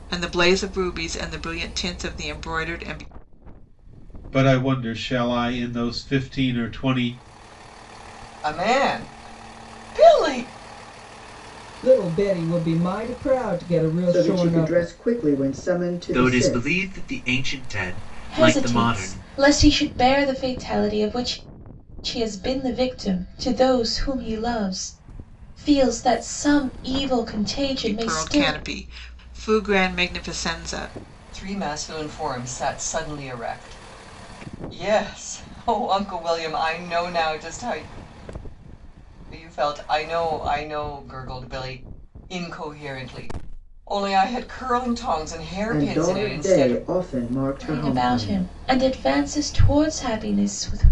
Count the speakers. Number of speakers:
7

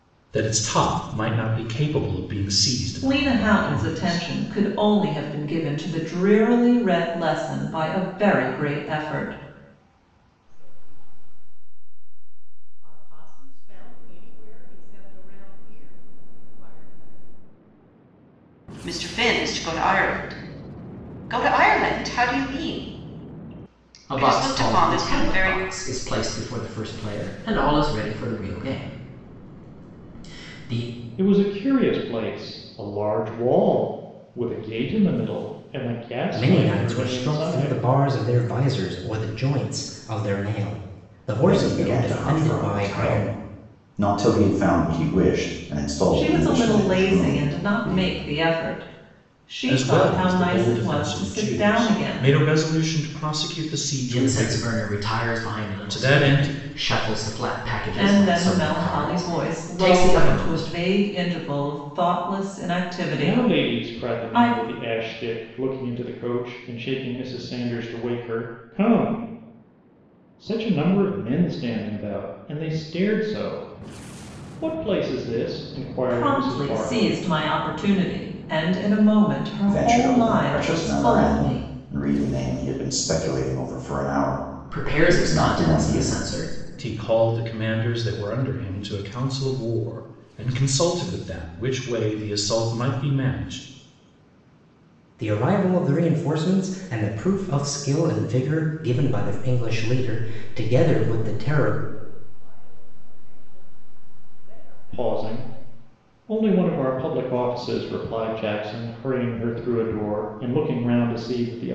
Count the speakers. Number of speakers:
8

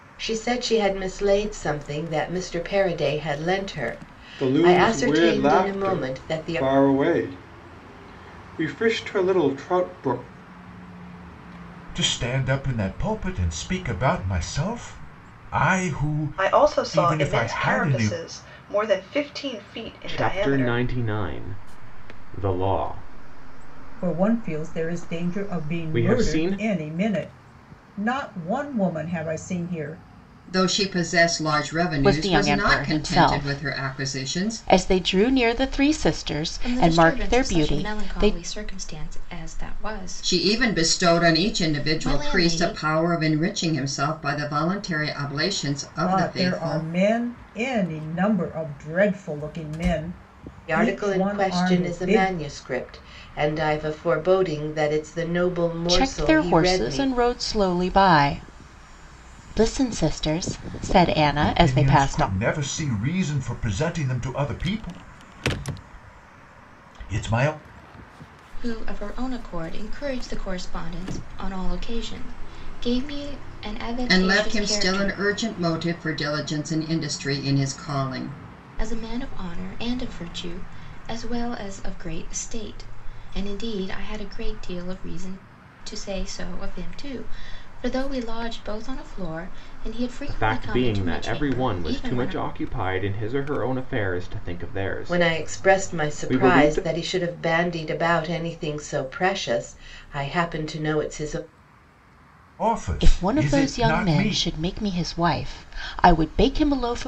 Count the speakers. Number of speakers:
9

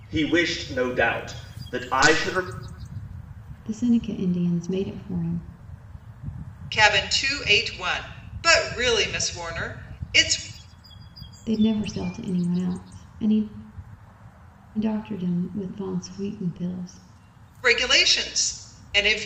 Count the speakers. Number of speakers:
3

